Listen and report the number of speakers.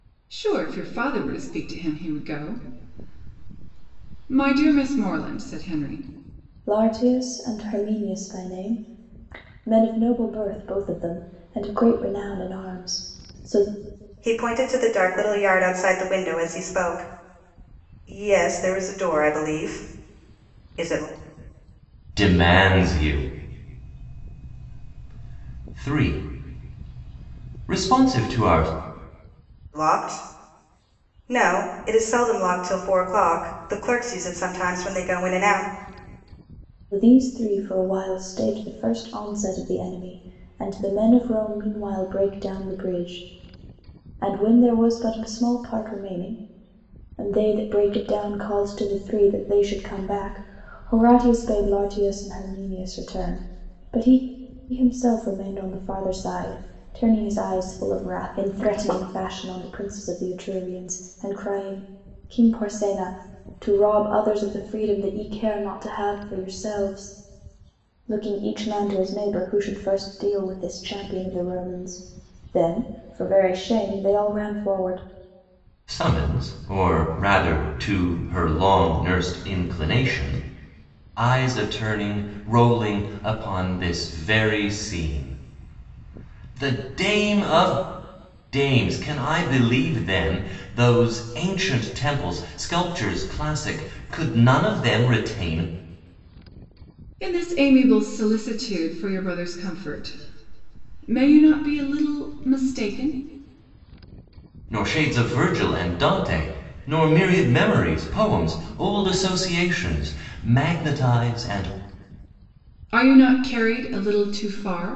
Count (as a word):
four